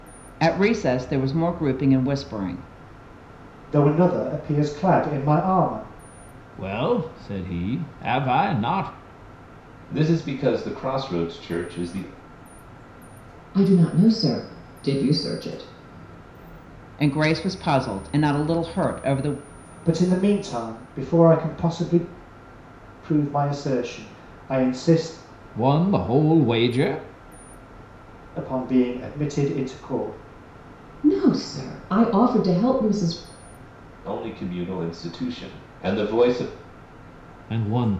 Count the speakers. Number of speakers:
five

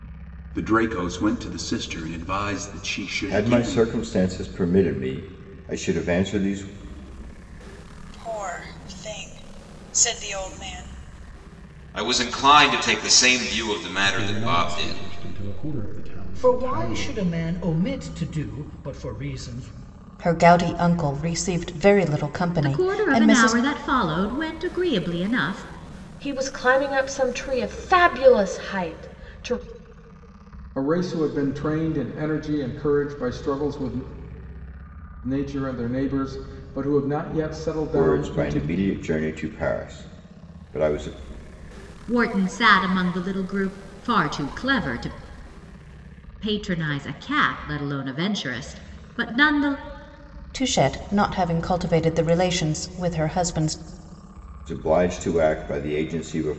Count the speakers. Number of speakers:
ten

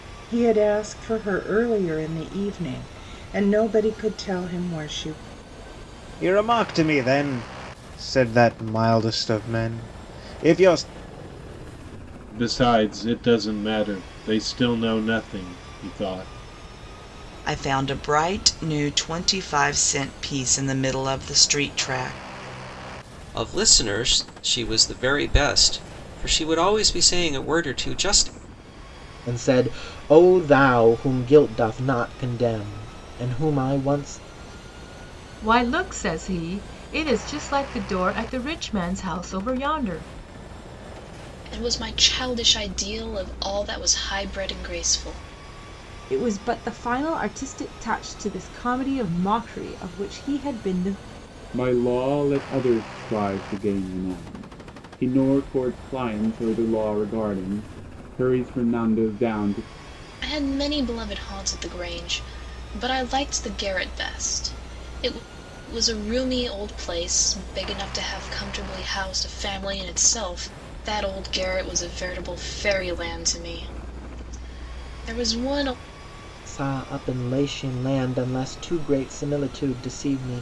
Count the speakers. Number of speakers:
ten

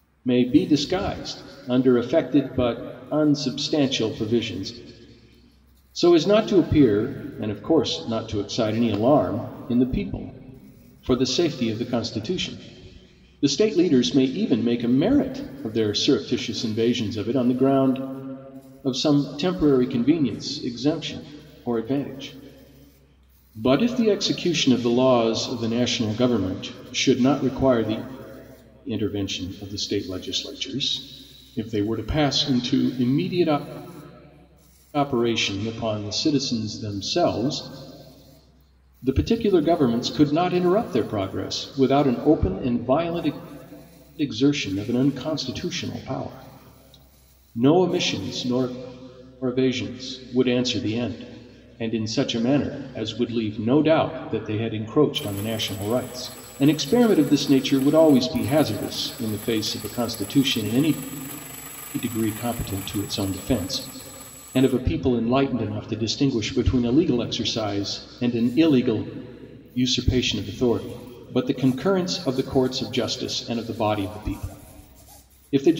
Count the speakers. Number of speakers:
one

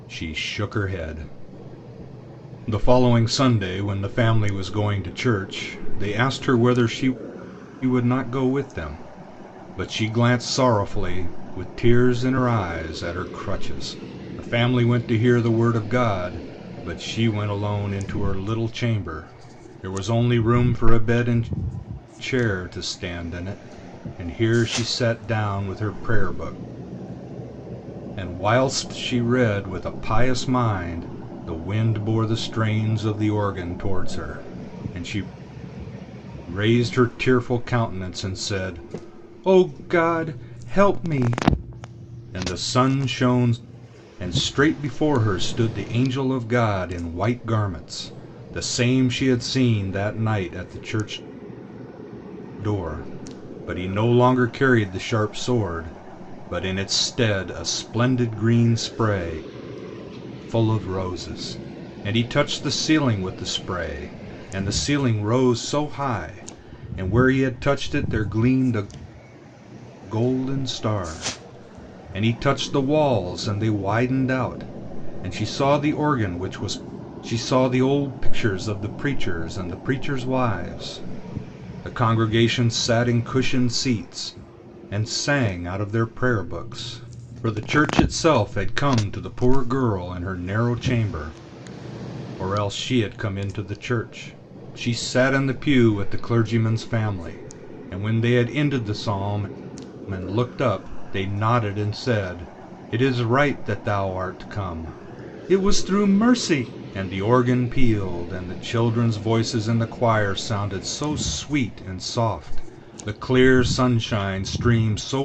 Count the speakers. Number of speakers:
one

